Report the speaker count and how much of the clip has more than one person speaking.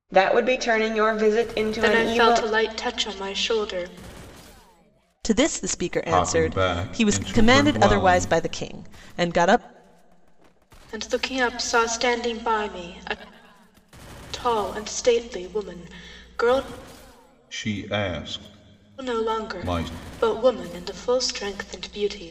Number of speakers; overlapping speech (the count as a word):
four, about 18%